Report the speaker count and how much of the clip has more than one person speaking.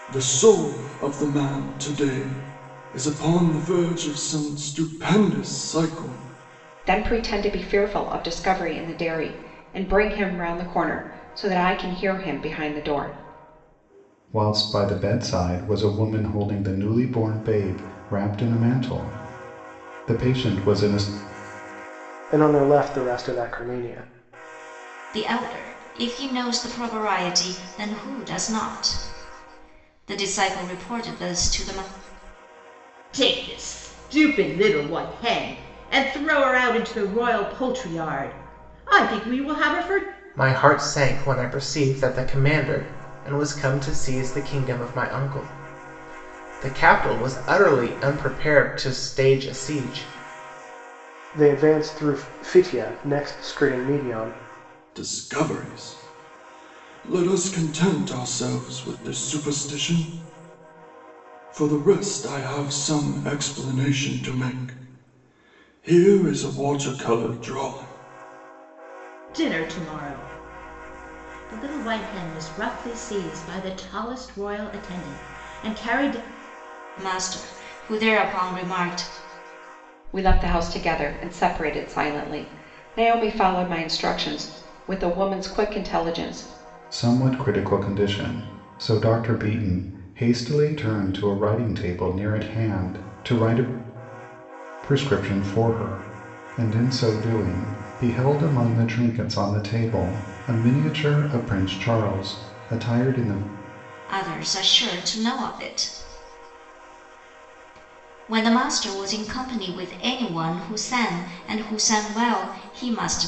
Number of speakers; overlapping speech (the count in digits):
7, no overlap